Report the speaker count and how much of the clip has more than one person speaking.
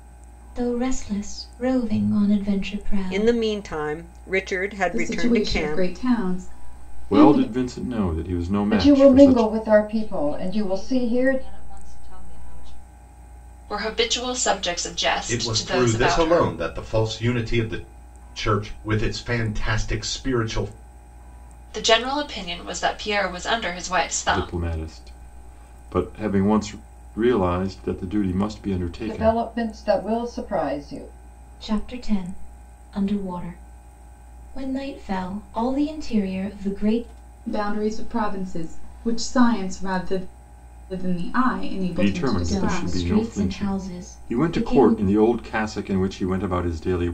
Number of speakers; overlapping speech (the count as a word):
eight, about 19%